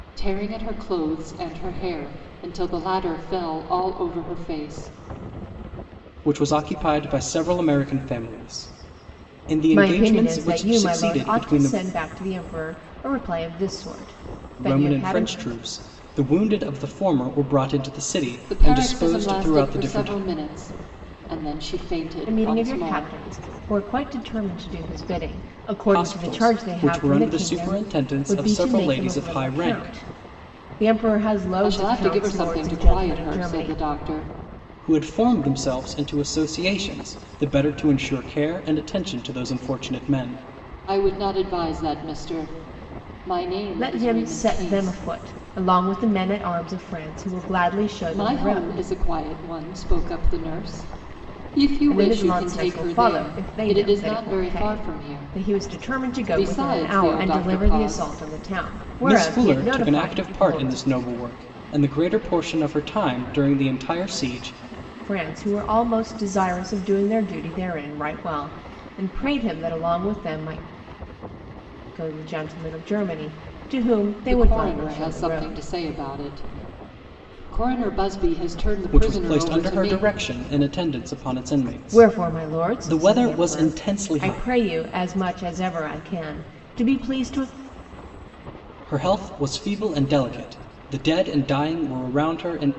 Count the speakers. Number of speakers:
3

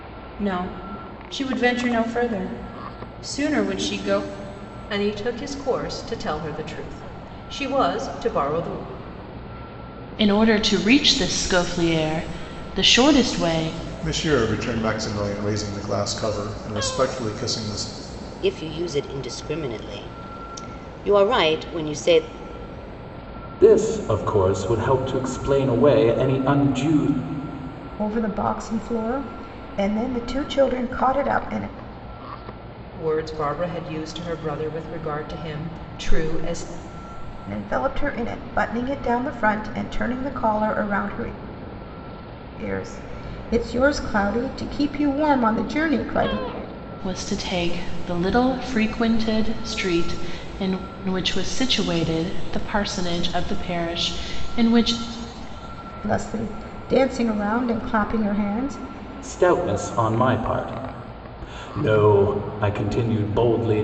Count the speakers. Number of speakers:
7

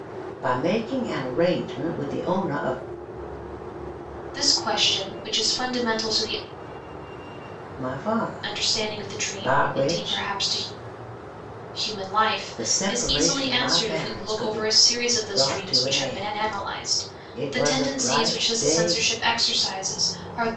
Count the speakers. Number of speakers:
2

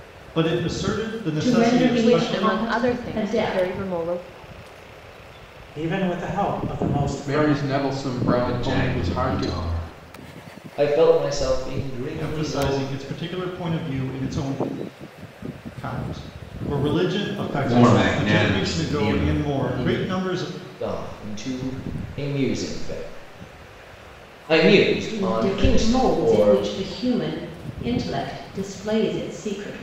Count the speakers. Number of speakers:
7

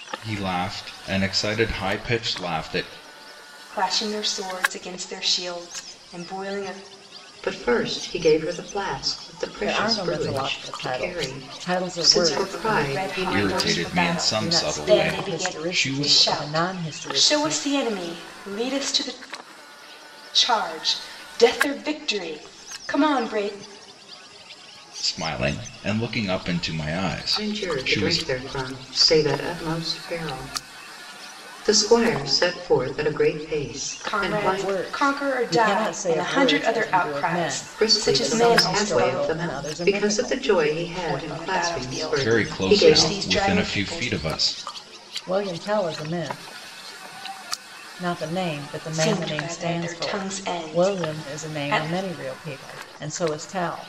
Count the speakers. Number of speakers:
4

